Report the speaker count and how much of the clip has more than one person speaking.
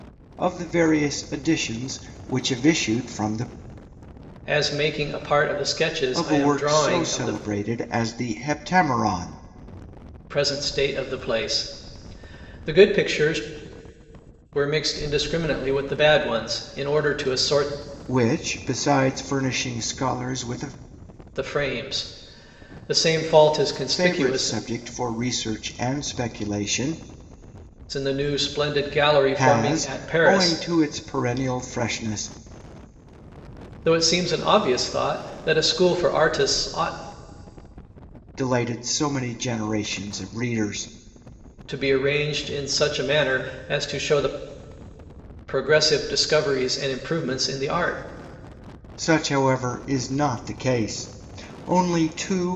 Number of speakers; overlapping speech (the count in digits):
2, about 6%